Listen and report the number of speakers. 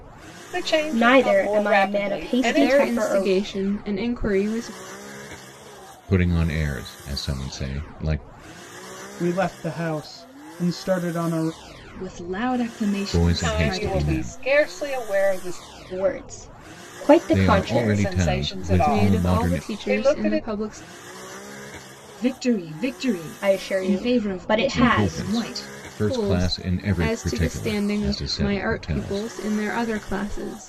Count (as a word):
six